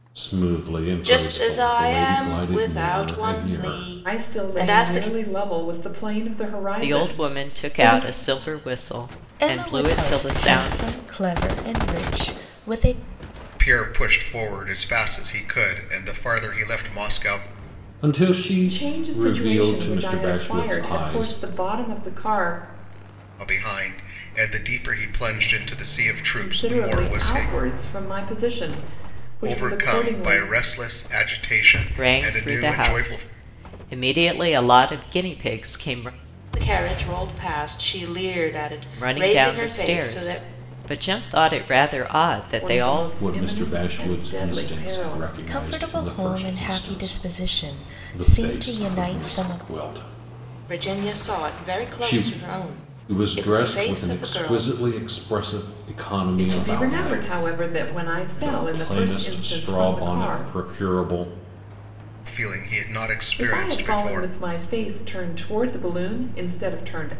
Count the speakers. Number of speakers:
six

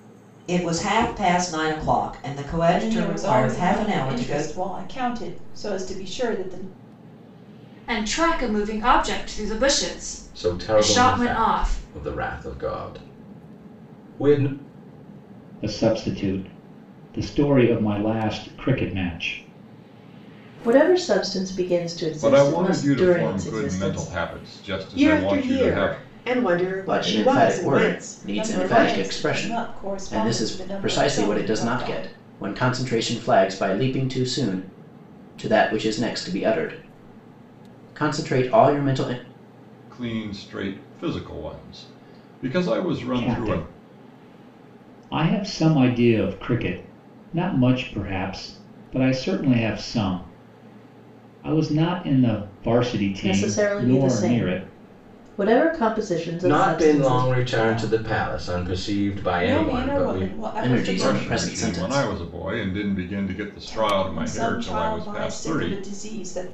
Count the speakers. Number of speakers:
nine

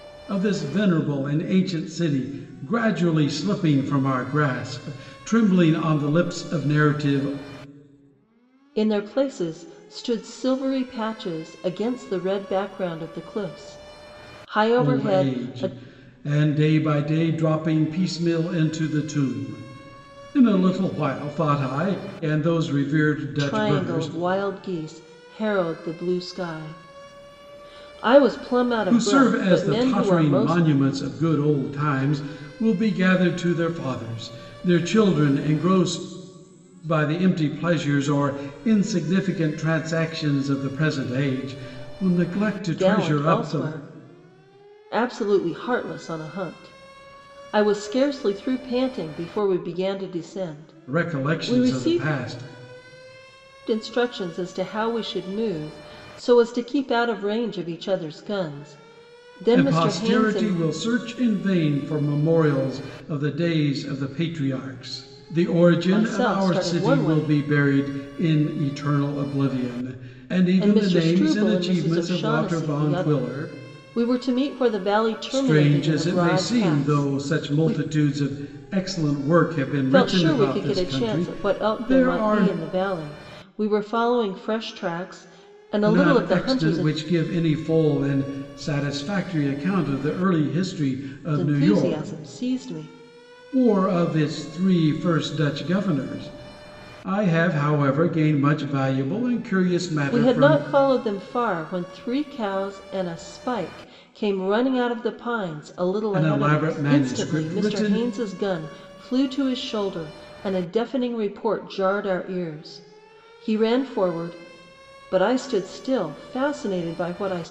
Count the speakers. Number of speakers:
two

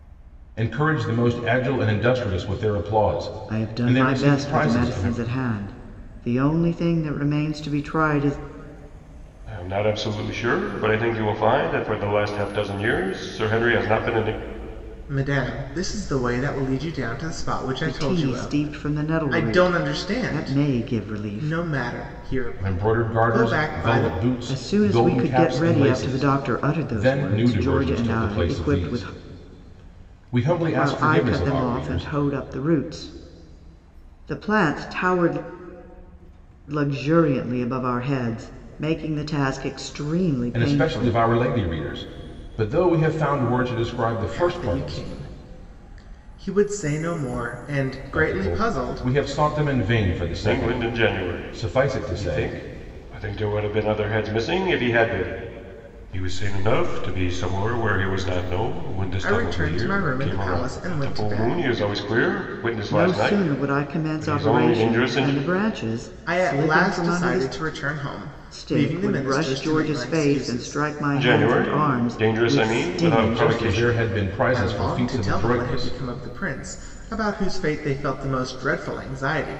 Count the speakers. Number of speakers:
four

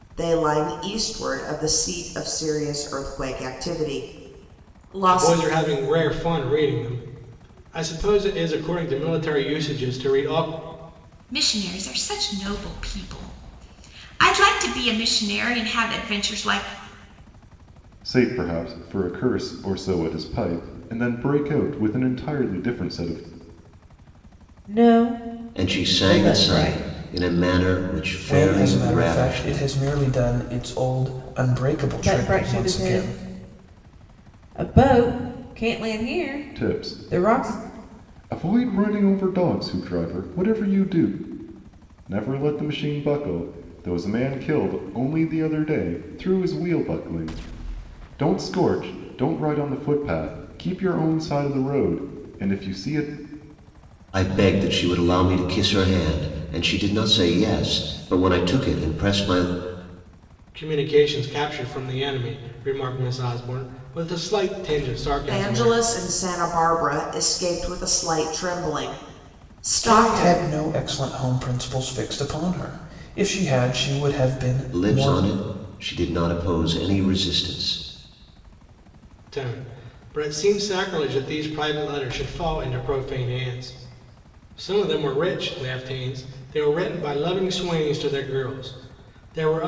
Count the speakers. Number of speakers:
seven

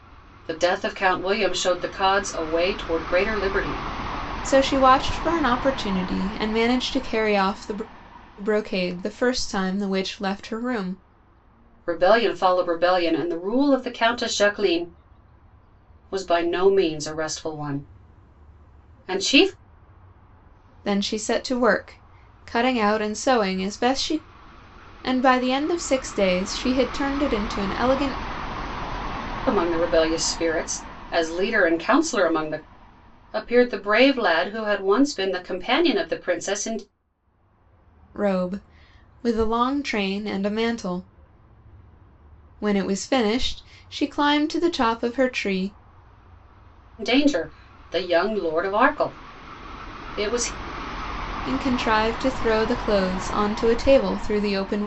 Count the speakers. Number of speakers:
two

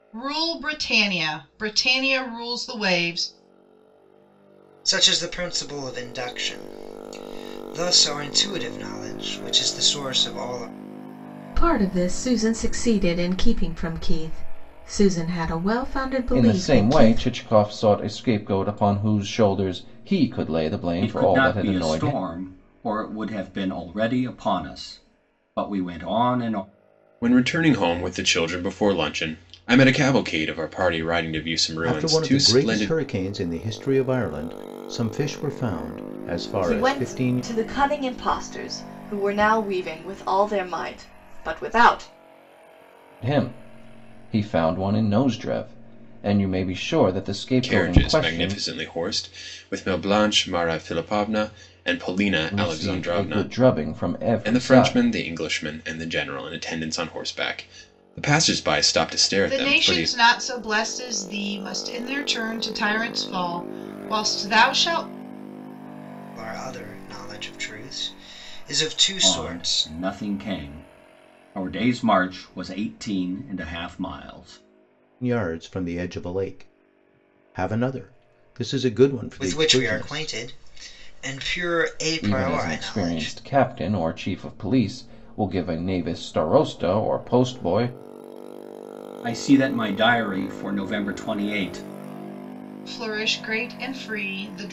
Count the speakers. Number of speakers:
eight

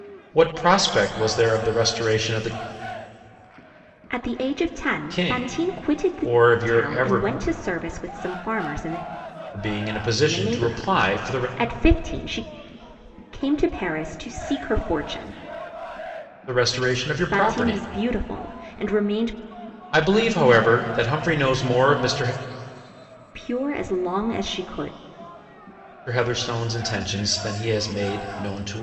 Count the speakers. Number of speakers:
two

